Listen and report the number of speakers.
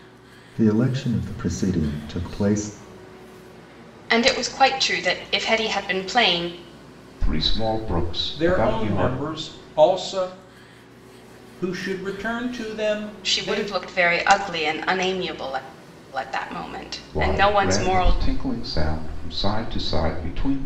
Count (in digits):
4